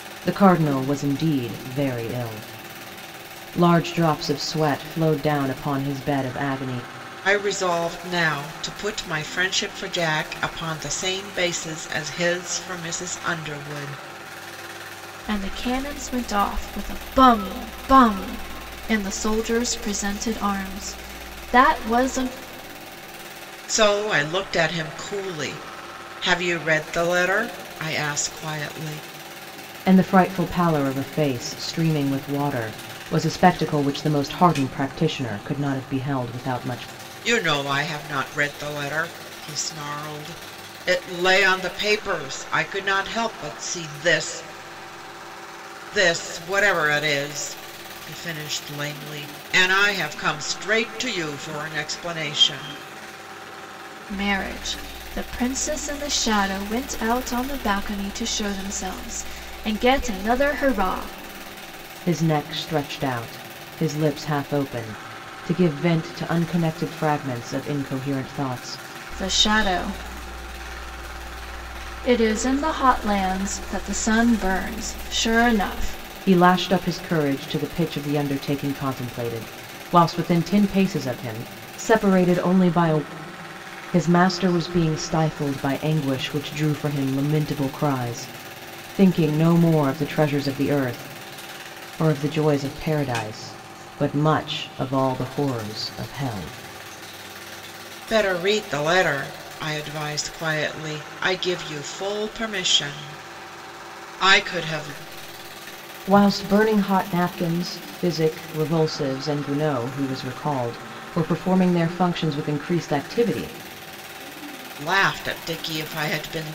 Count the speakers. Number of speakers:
3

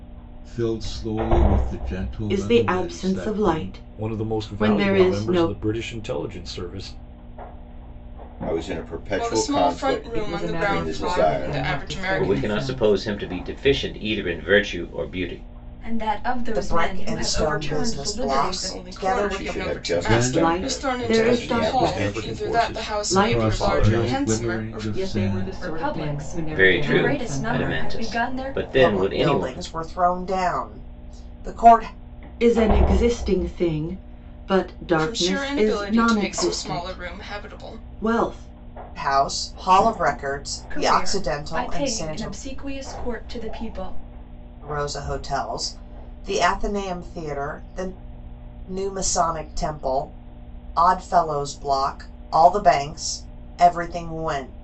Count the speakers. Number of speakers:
9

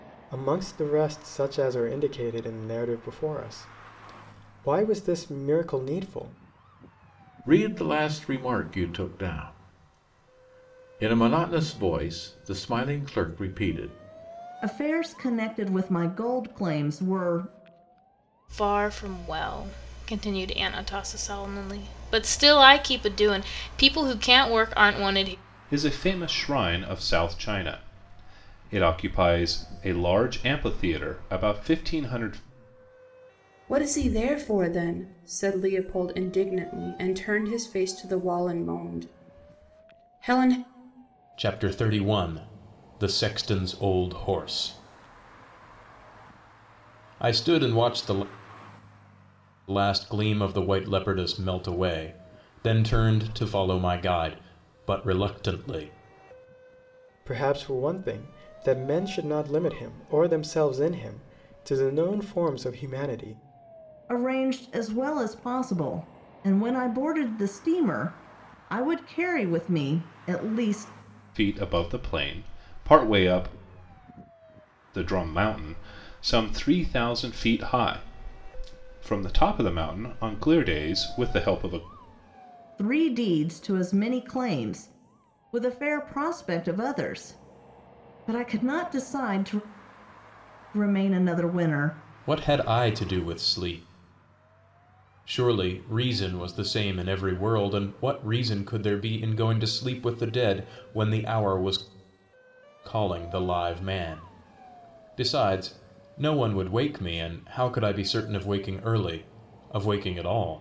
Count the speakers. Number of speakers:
7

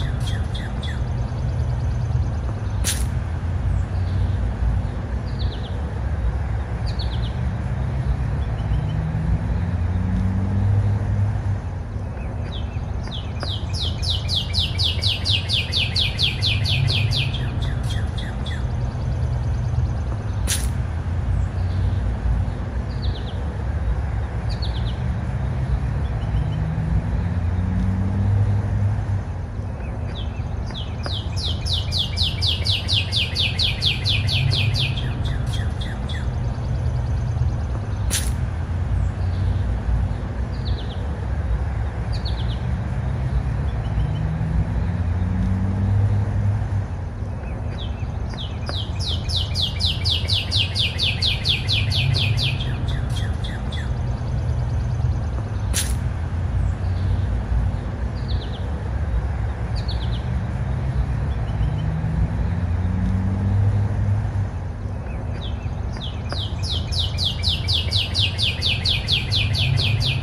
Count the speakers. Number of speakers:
0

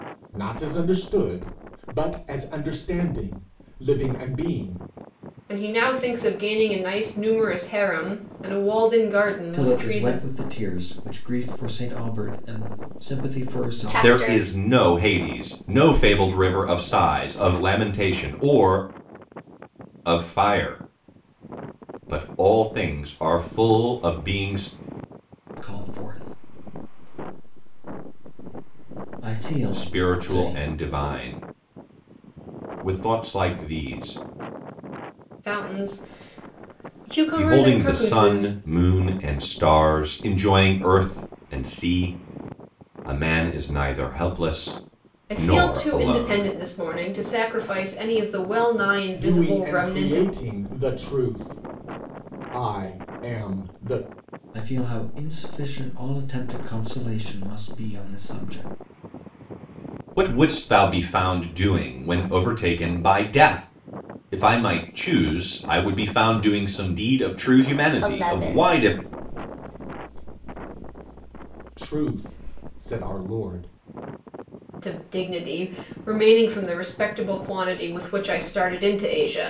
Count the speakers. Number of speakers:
5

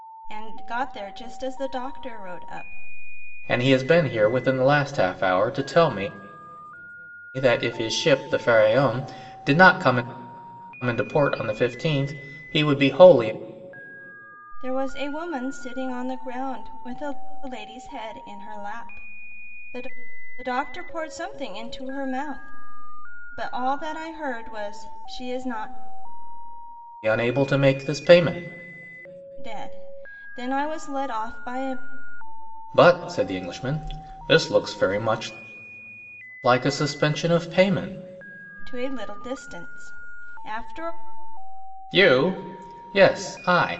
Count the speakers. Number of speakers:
2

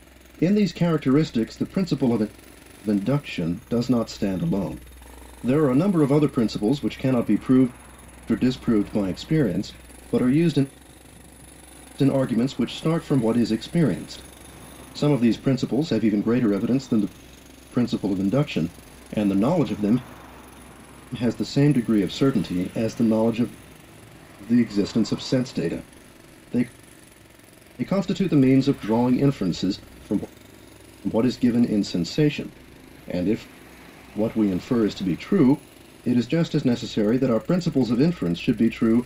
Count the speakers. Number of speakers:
1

